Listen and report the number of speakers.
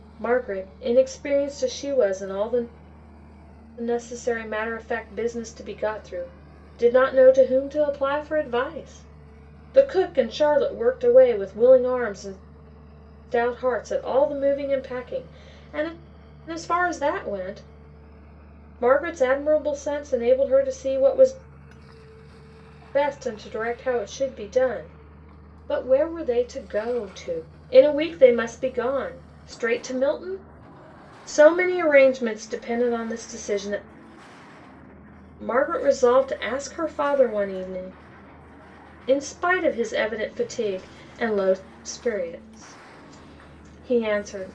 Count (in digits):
1